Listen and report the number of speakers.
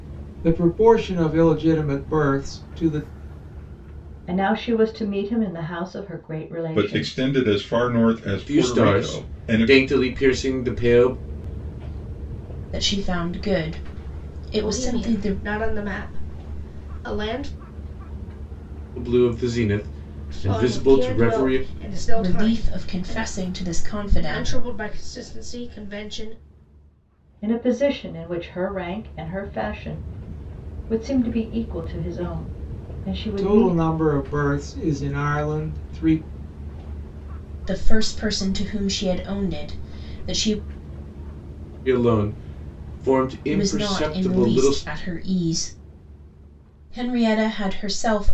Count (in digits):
6